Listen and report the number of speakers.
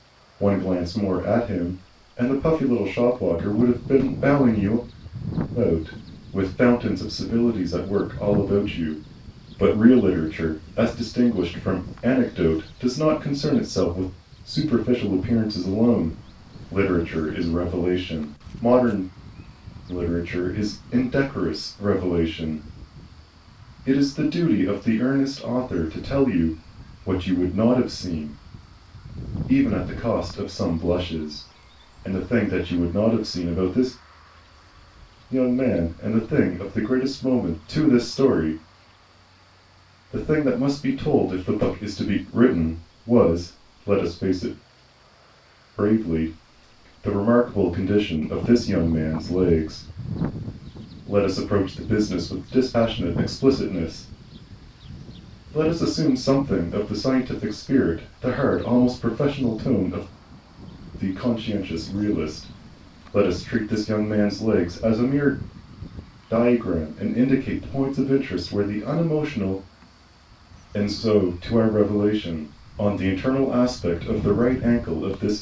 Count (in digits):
1